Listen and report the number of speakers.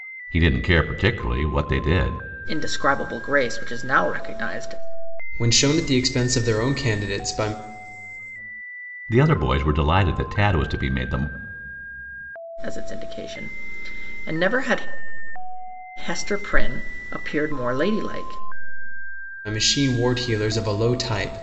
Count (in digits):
3